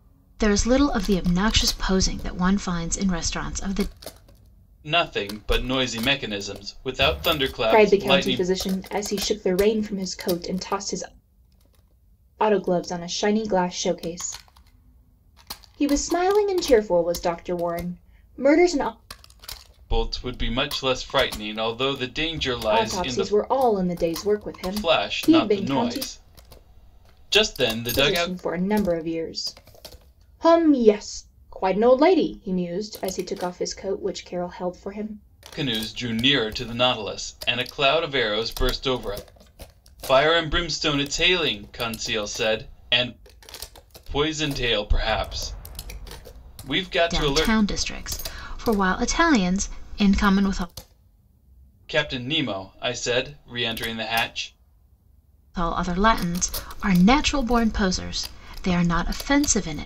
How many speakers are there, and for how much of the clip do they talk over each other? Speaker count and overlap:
three, about 7%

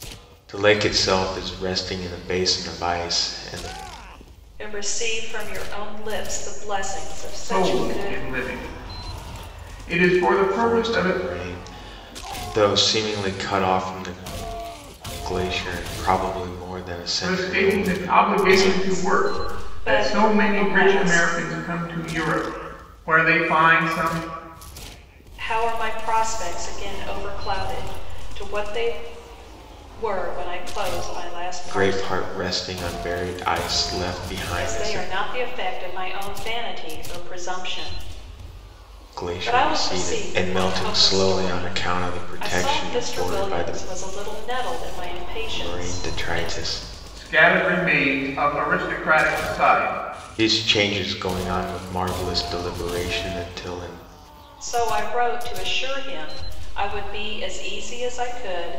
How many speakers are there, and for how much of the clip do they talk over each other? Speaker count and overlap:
three, about 21%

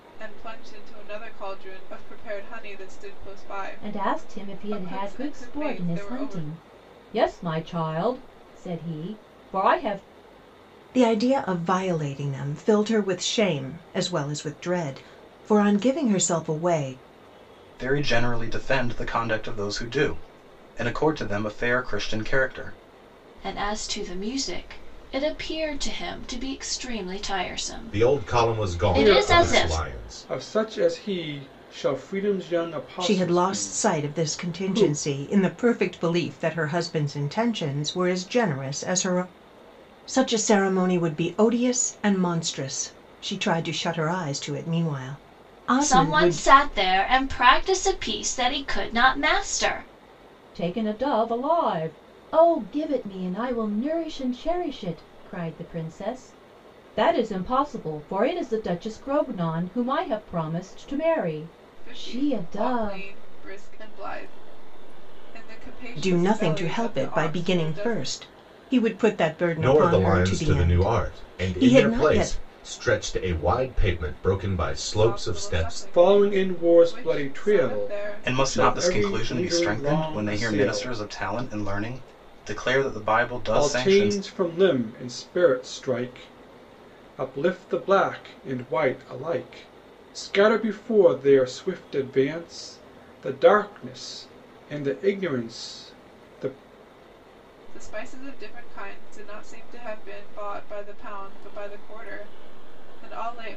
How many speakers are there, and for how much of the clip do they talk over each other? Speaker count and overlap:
seven, about 20%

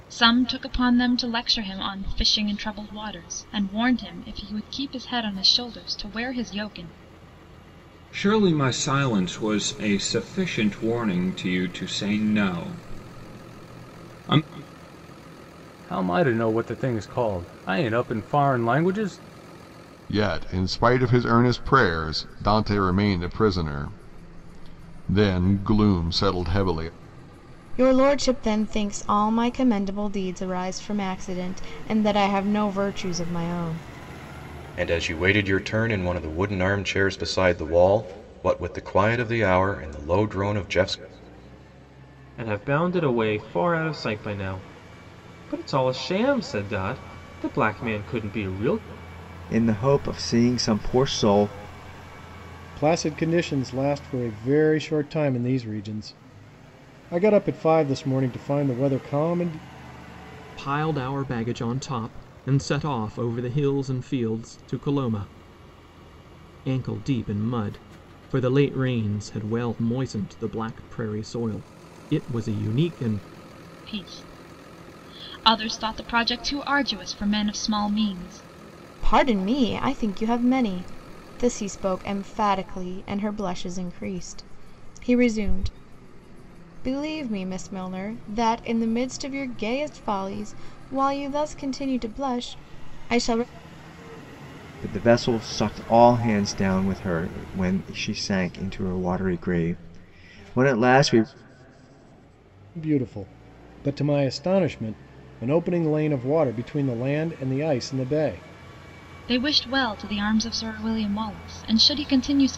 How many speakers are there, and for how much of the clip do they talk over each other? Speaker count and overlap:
ten, no overlap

